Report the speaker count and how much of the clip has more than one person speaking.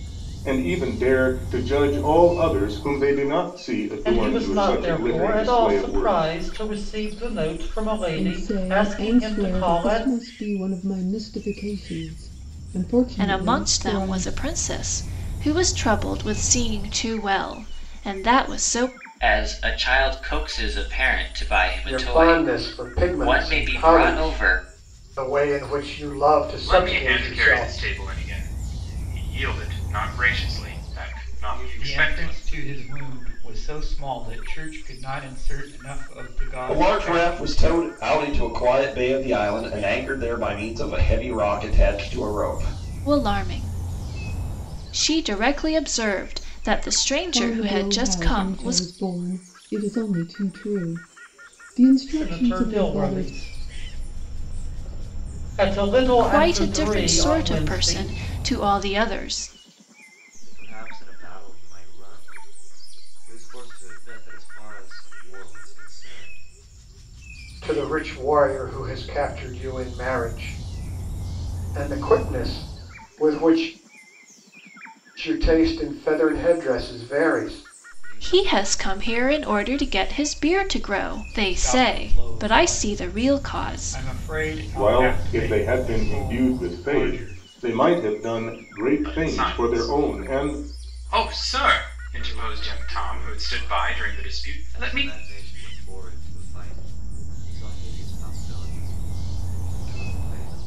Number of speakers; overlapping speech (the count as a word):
ten, about 29%